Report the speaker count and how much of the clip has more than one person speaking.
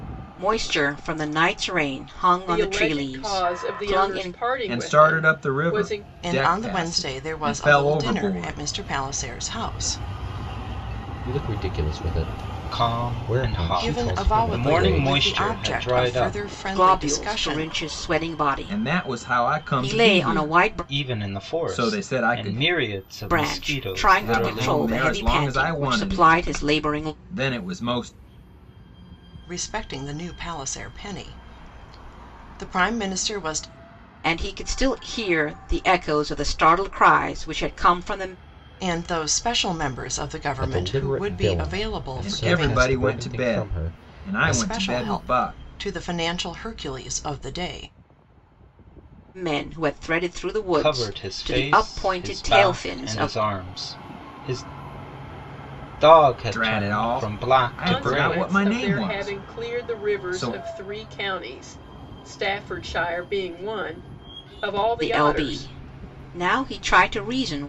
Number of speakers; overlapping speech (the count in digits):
6, about 46%